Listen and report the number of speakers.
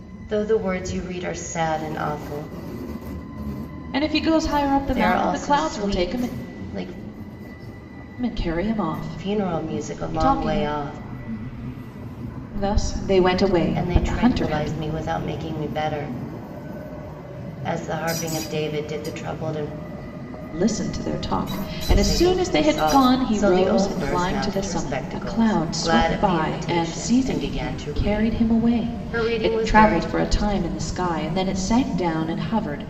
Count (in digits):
2